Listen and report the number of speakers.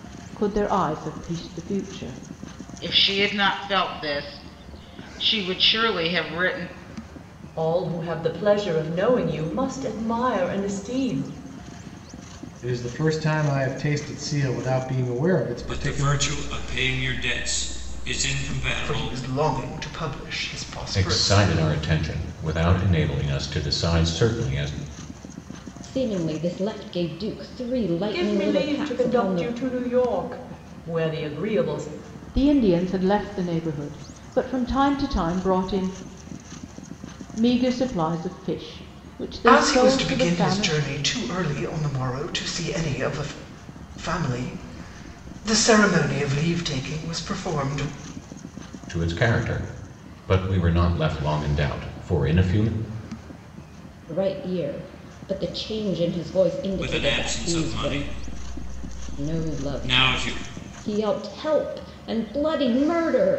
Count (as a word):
eight